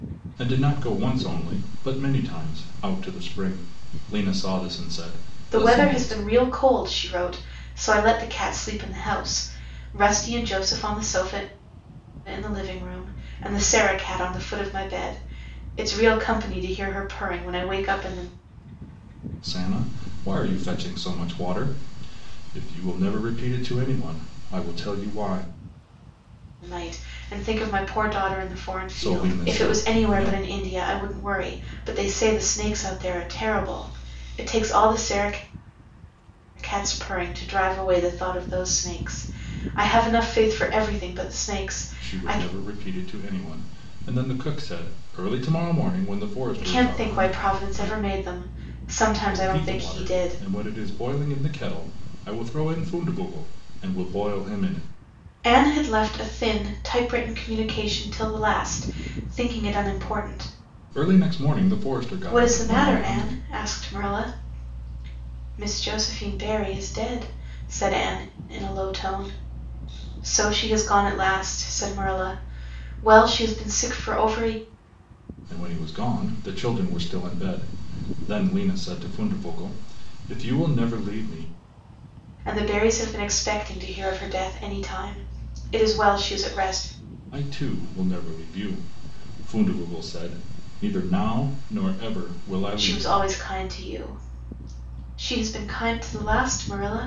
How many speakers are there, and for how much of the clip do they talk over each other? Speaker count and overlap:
2, about 7%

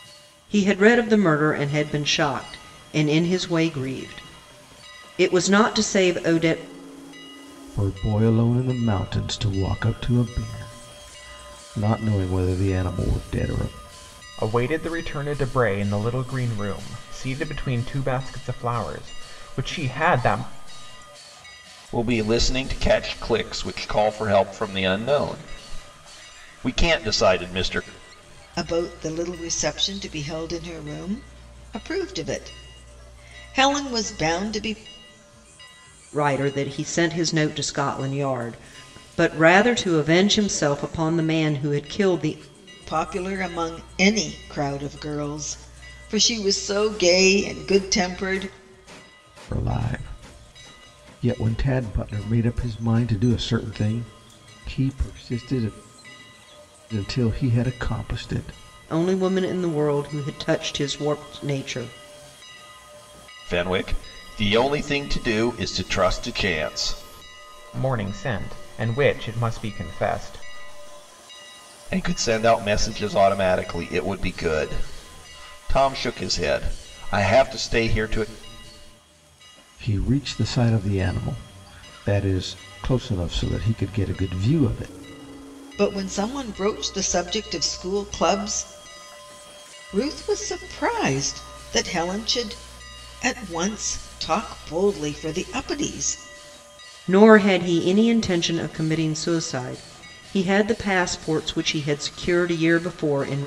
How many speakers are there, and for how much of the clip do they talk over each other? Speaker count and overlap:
5, no overlap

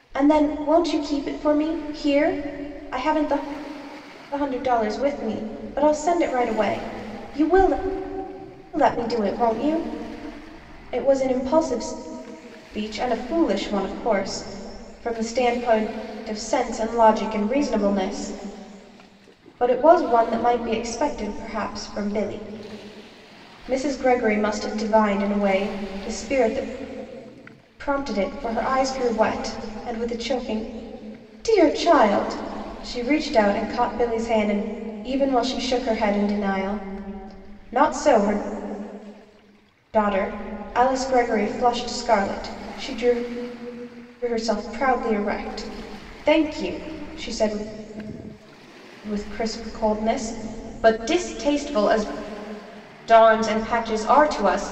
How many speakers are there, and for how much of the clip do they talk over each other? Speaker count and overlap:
1, no overlap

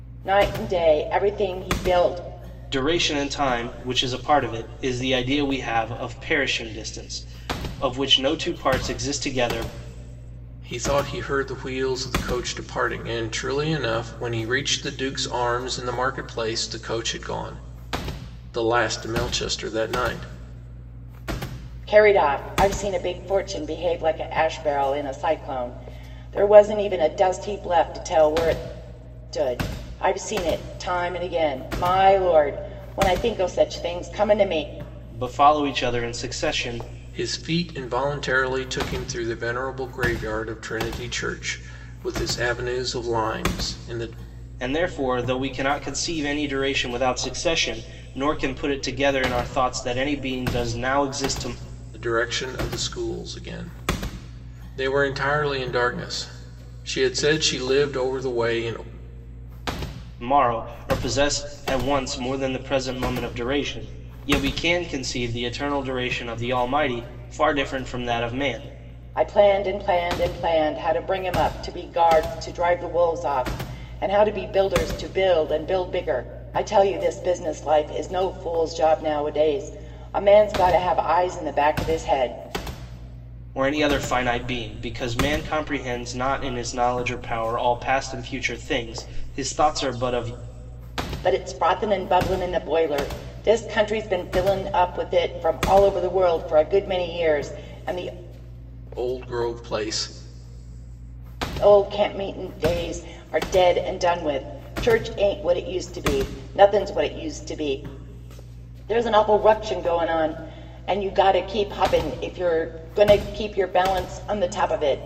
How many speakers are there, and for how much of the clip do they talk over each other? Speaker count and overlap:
3, no overlap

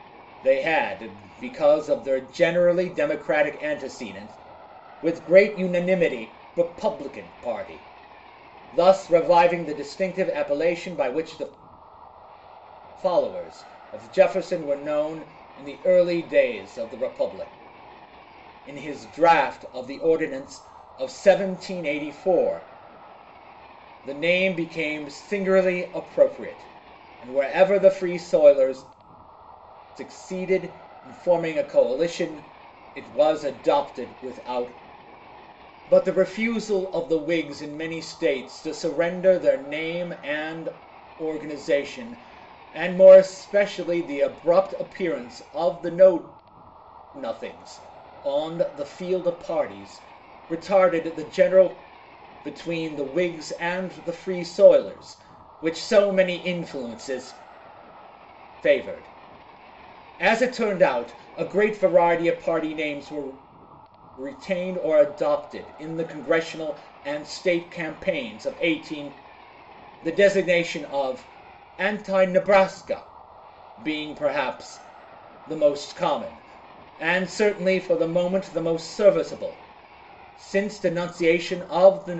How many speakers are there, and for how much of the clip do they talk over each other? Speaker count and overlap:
1, no overlap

